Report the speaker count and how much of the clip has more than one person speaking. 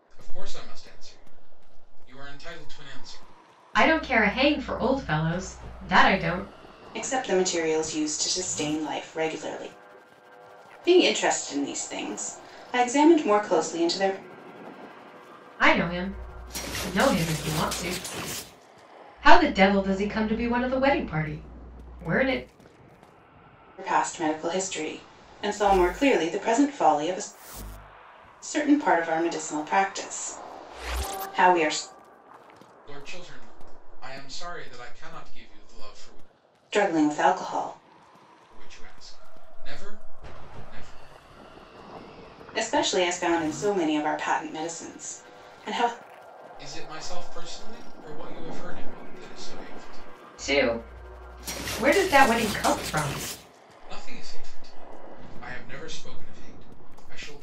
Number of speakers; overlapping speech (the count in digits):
3, no overlap